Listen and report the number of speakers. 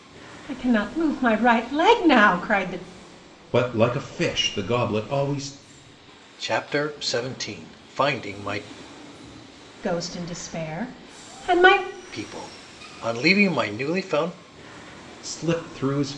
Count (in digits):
3